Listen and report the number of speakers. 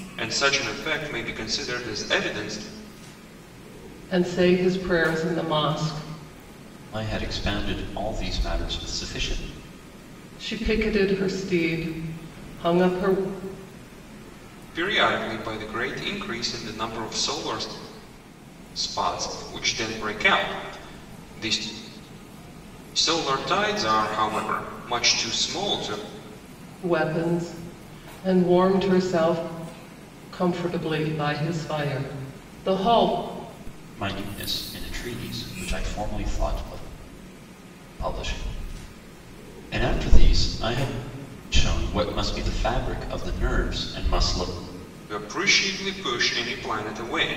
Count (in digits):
3